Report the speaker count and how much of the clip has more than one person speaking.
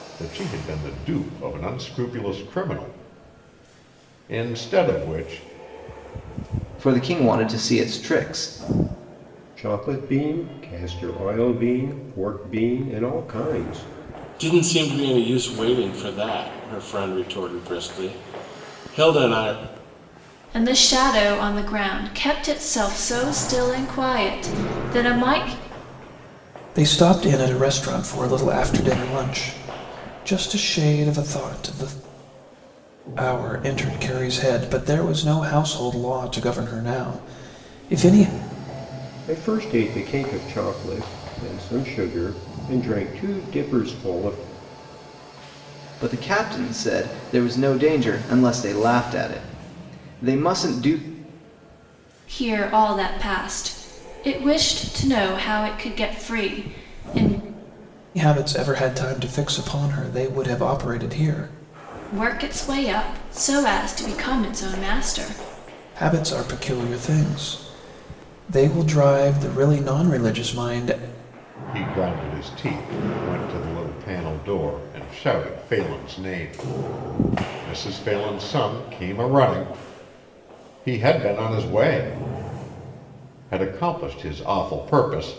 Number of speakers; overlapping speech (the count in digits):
6, no overlap